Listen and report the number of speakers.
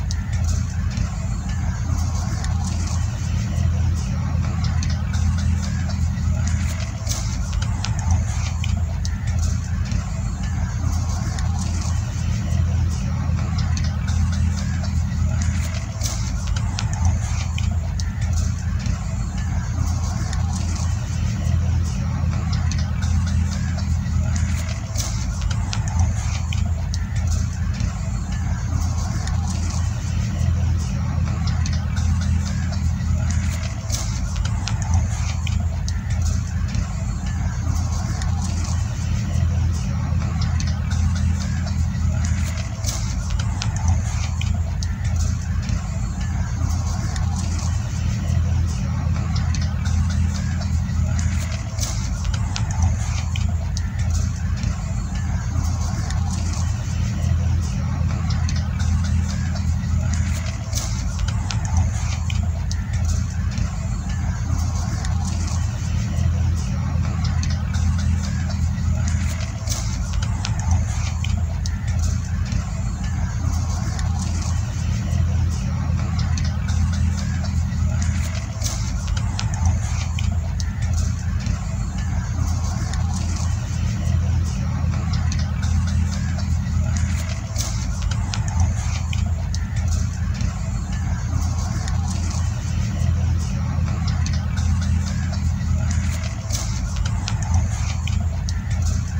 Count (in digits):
0